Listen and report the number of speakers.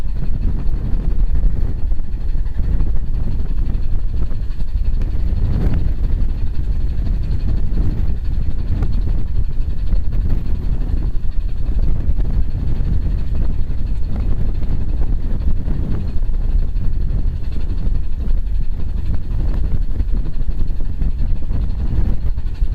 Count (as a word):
zero